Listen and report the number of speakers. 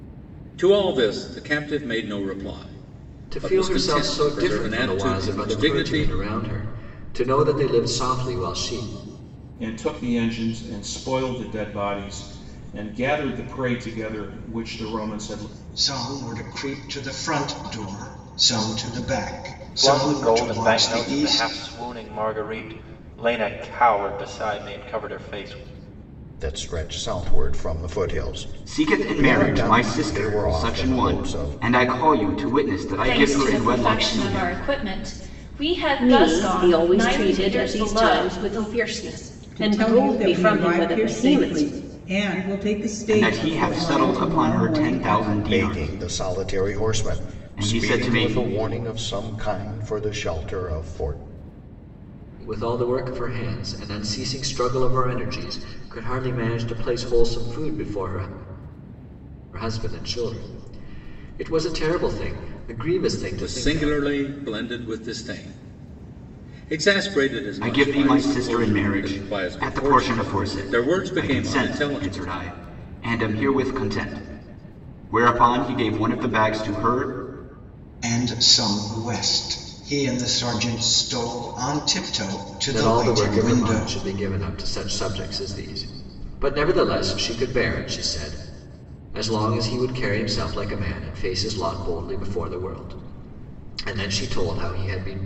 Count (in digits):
10